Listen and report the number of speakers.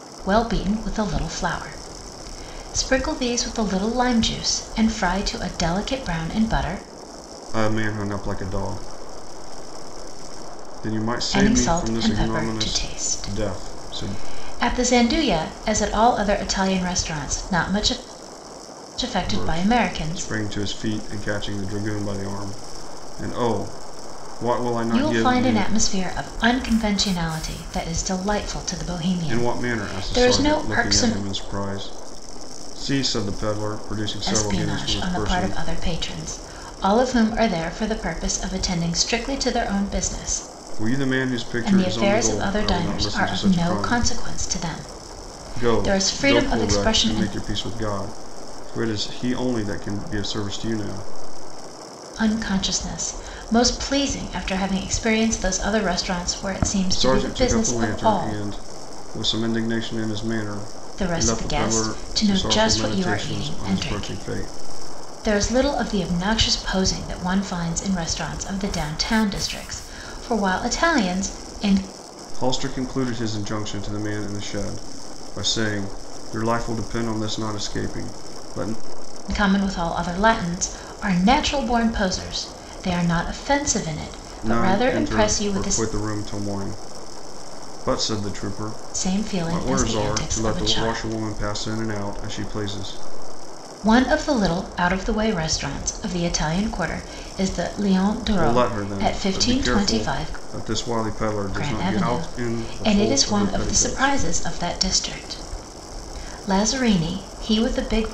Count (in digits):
2